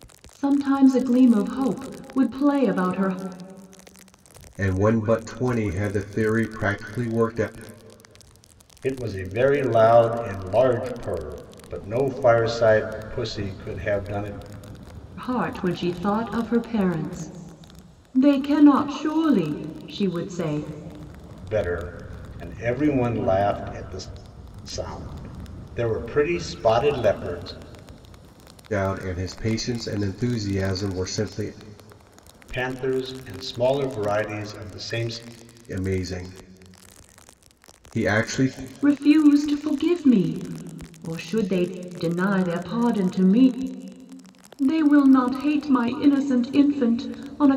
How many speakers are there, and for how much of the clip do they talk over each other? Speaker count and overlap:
three, no overlap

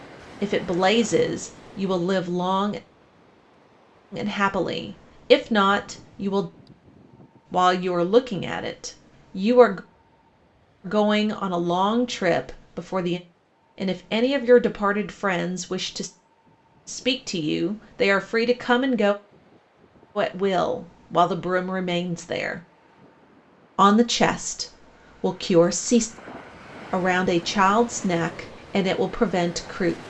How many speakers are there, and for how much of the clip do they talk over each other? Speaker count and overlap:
one, no overlap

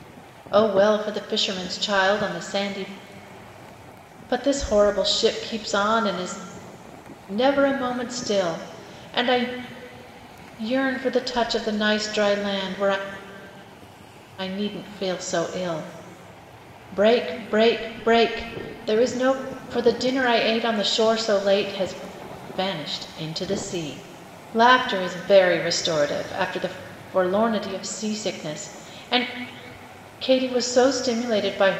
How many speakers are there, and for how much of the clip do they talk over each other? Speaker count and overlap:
one, no overlap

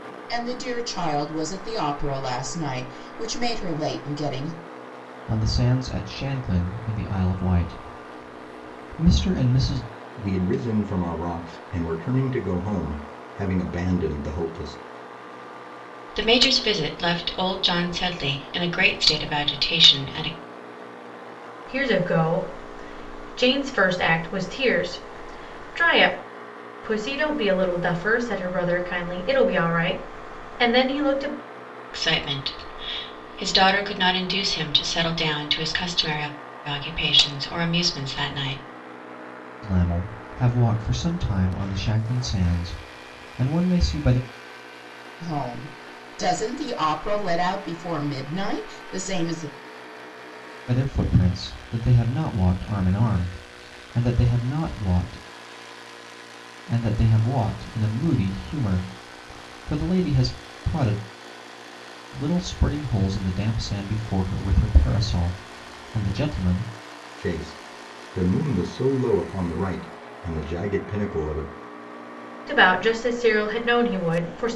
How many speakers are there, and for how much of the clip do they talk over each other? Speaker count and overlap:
five, no overlap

